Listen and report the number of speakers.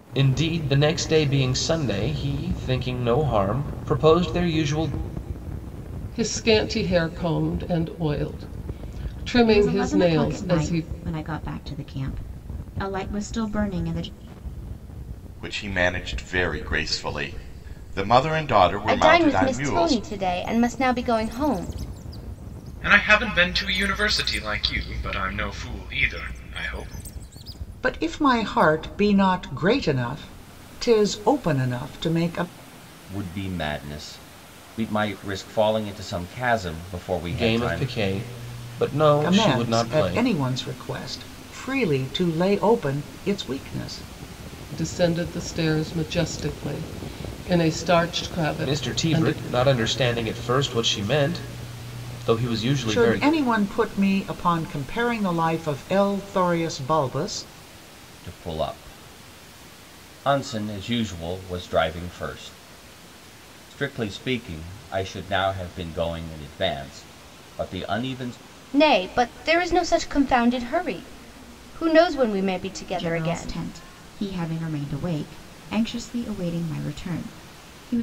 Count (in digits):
8